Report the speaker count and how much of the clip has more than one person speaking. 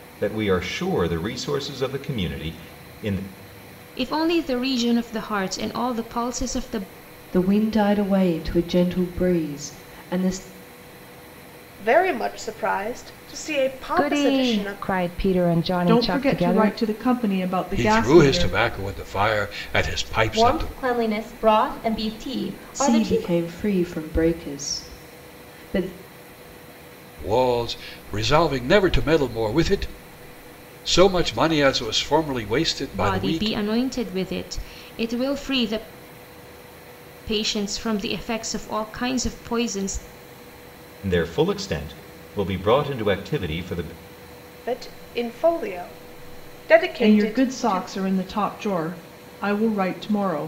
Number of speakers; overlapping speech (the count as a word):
eight, about 11%